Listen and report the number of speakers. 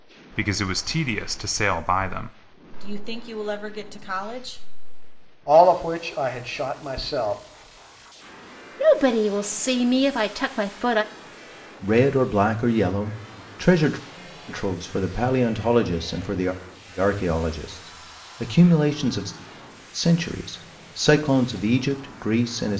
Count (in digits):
5